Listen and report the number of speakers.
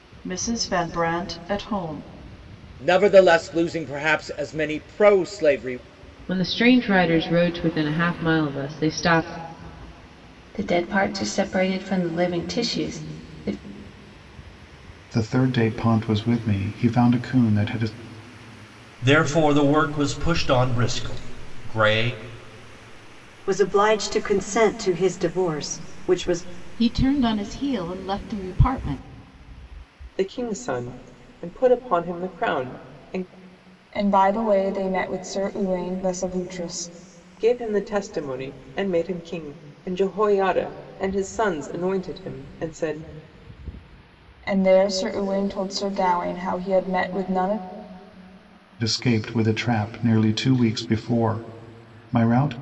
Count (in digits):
10